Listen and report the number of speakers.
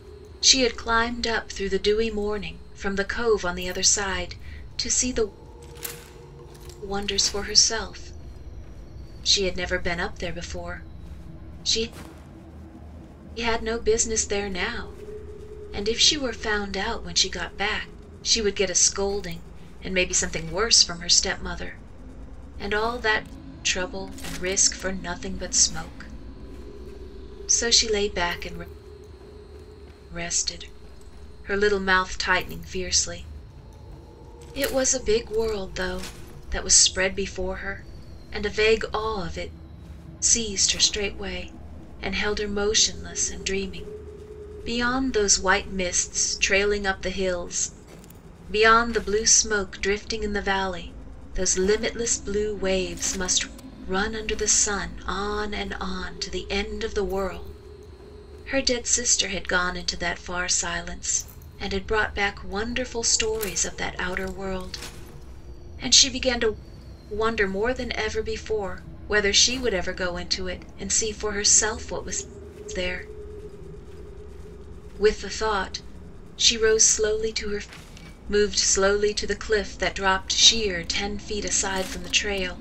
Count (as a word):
one